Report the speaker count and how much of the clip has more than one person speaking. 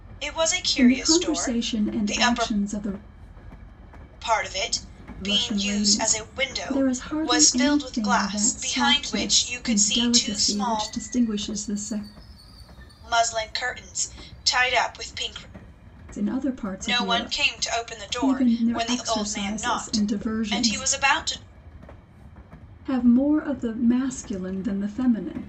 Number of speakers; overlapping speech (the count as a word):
two, about 46%